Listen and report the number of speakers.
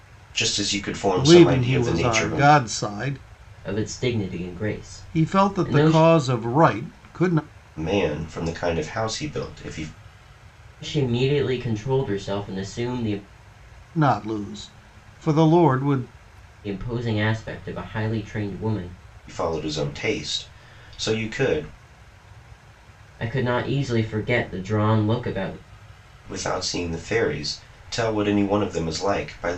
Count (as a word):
three